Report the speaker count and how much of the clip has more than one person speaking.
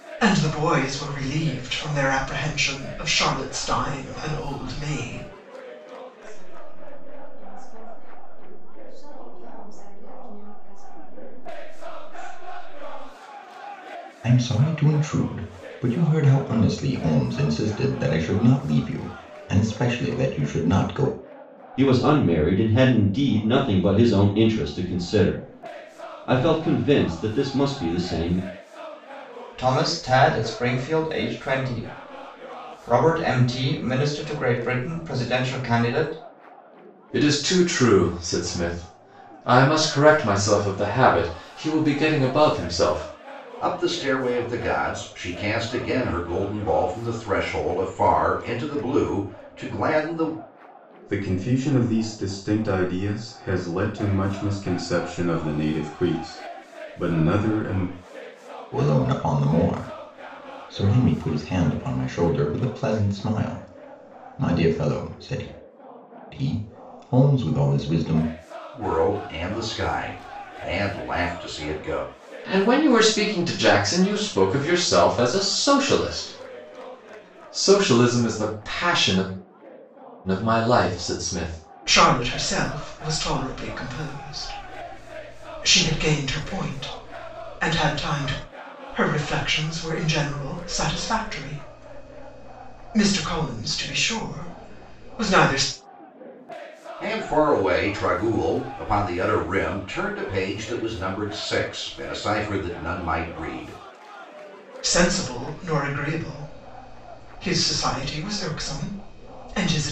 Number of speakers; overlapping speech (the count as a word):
eight, no overlap